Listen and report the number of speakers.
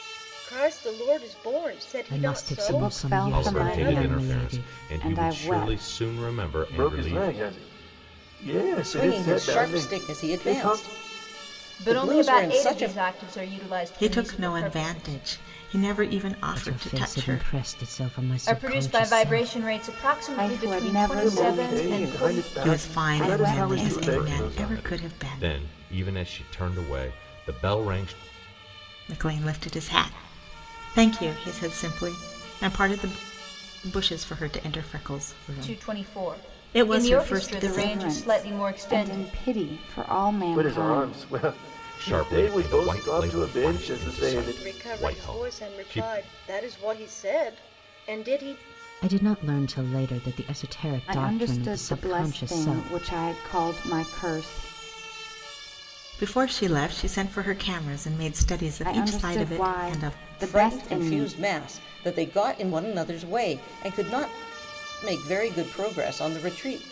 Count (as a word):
eight